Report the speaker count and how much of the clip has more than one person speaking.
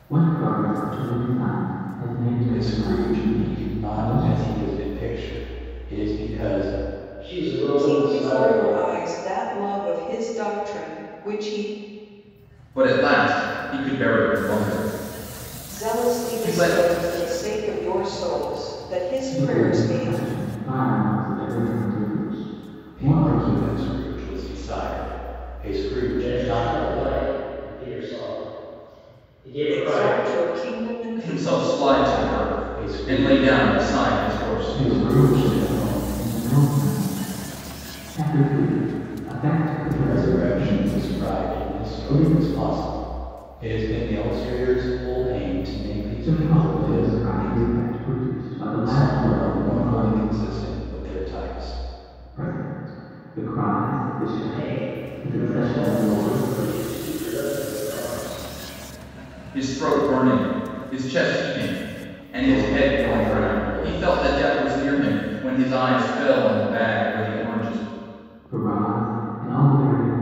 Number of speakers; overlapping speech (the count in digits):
5, about 31%